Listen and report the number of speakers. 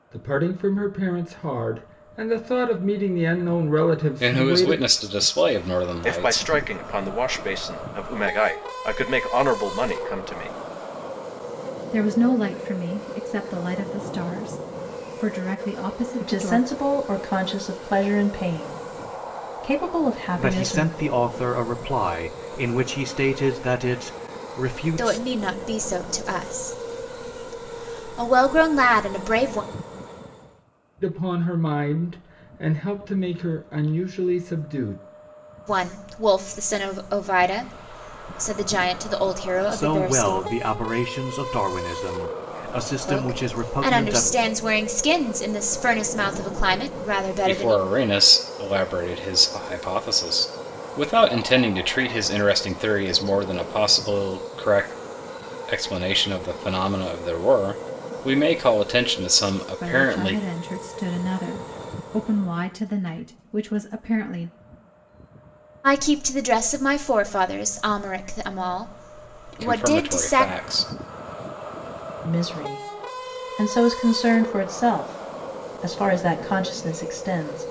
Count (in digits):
7